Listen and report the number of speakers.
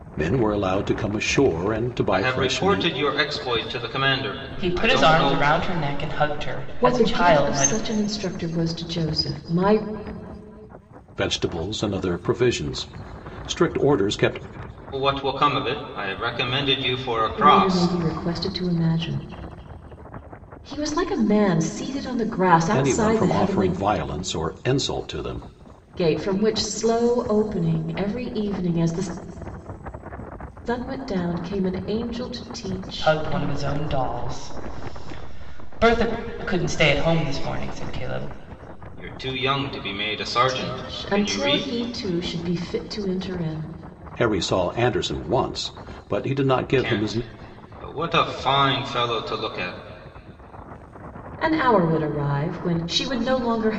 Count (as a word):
four